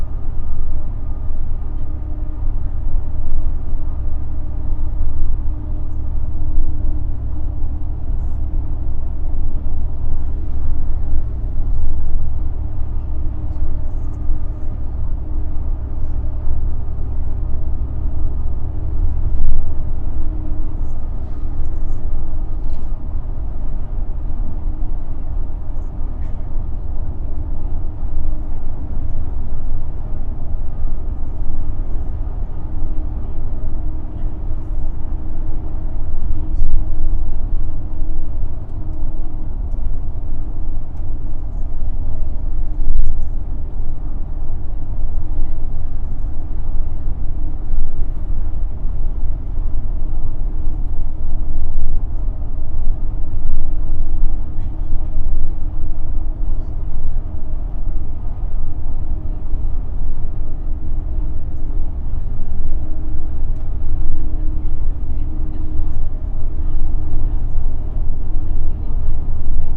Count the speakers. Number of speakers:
0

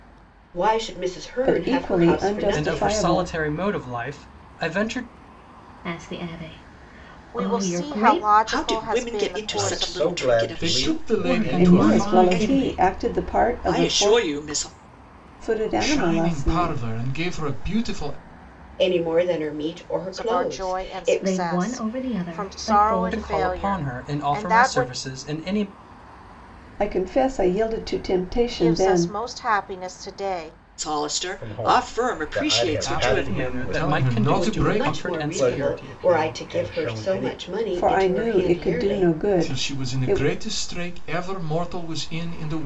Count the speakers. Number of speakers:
8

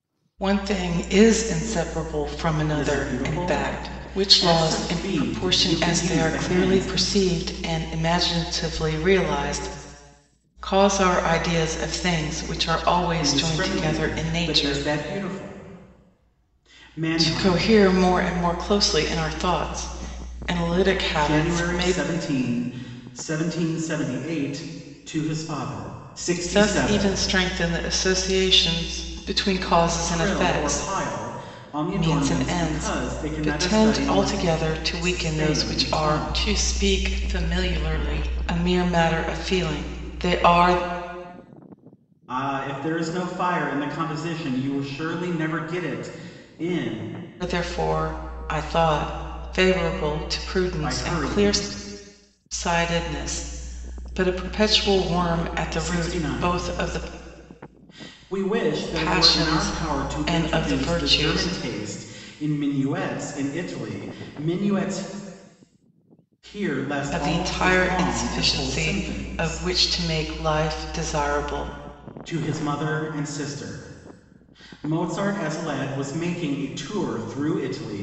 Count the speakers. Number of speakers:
2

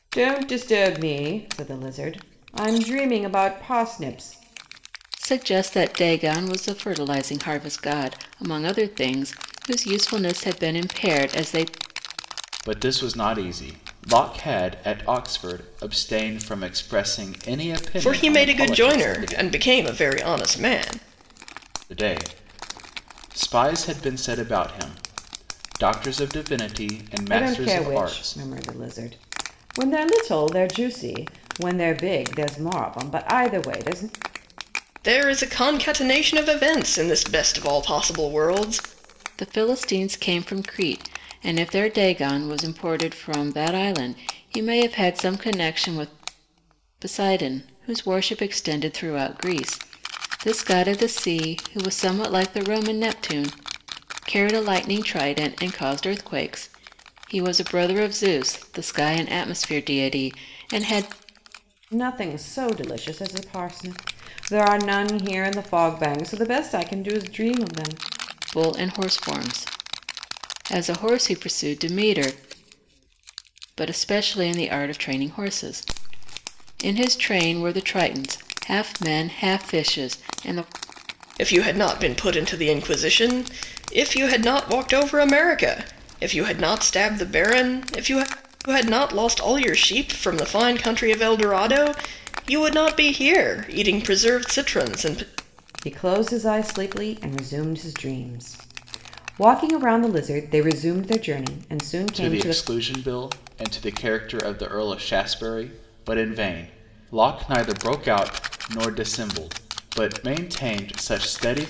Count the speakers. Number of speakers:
4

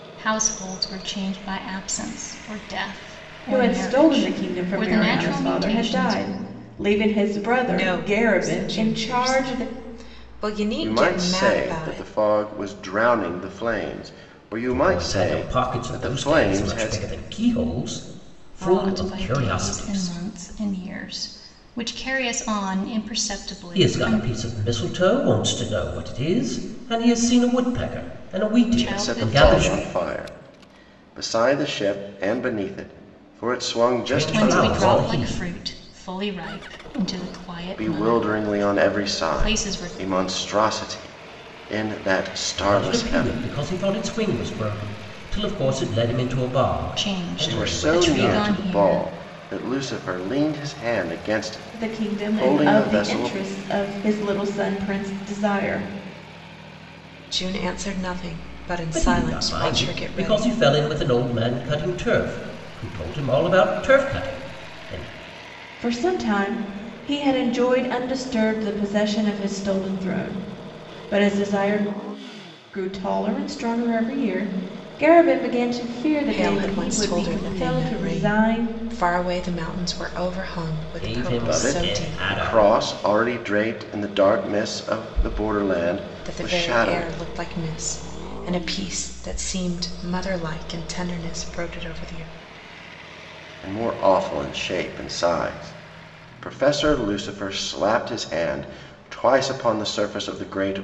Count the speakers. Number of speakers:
5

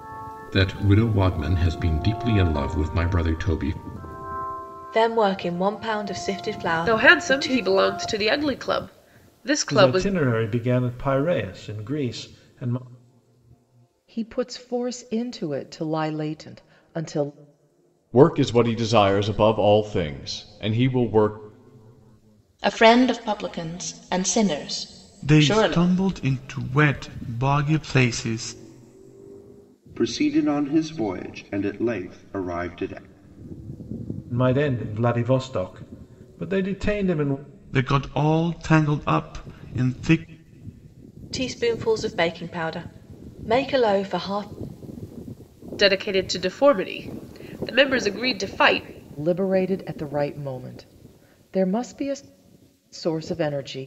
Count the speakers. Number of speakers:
9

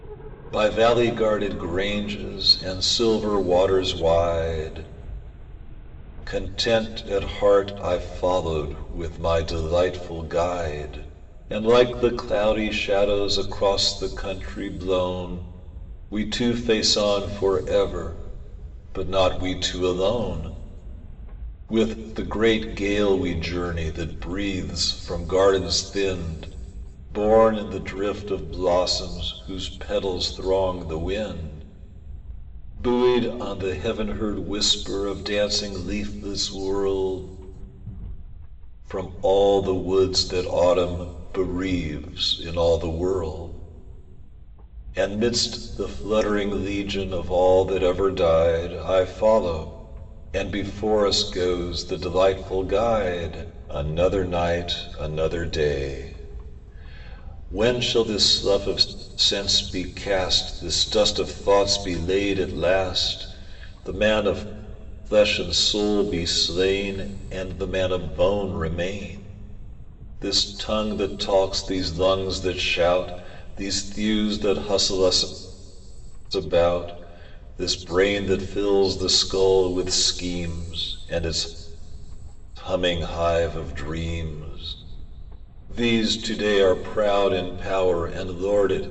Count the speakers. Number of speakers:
1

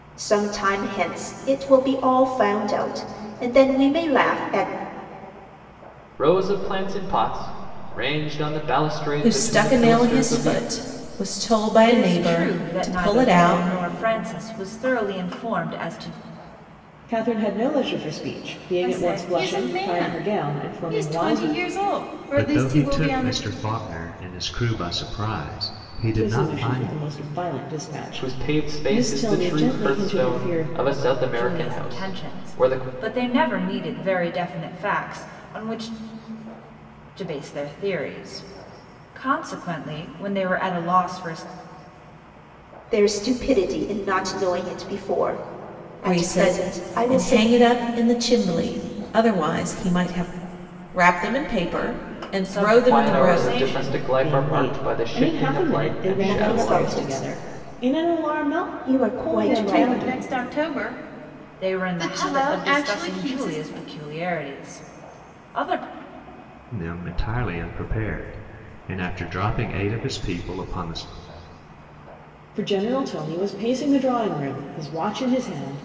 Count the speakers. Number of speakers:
7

